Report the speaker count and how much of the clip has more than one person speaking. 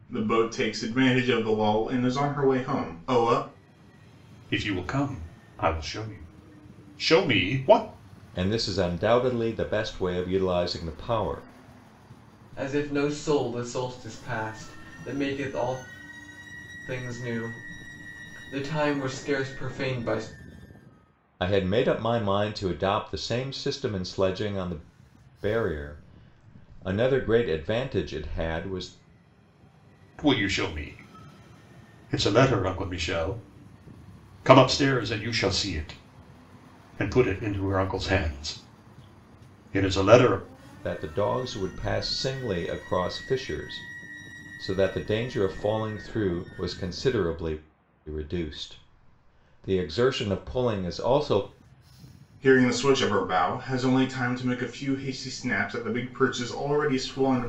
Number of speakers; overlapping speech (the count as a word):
four, no overlap